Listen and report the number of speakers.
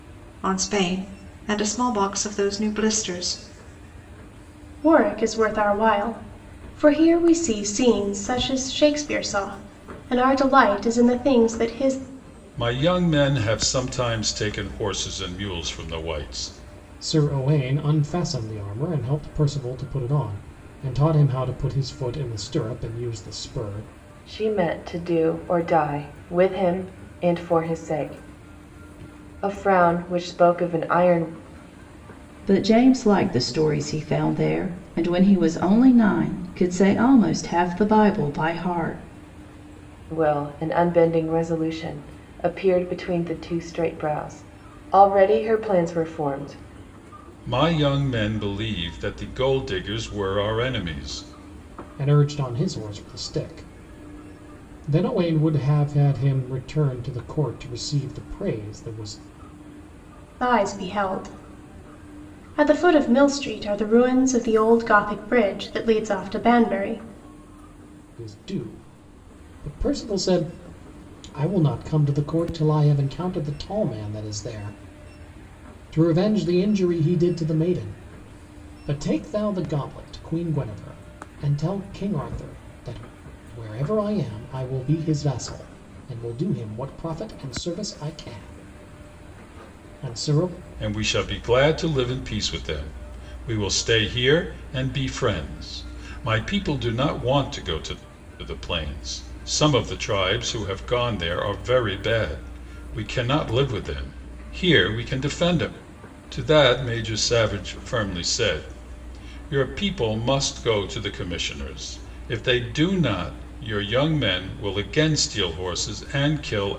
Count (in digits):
6